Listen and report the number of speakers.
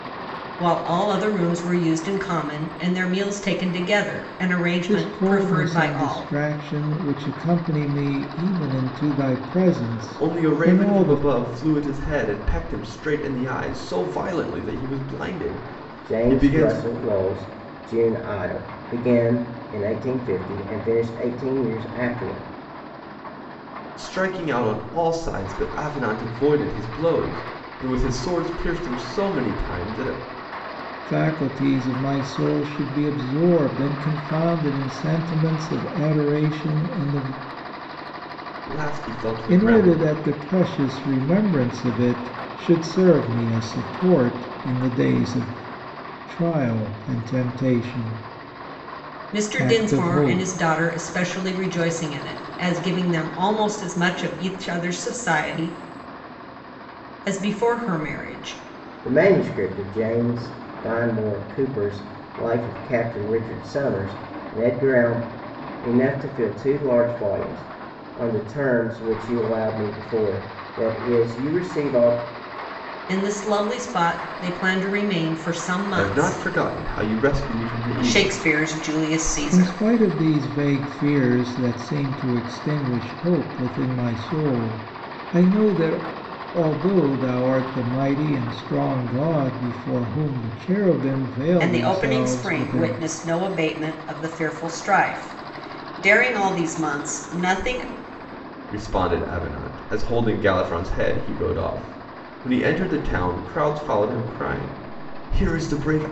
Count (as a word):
four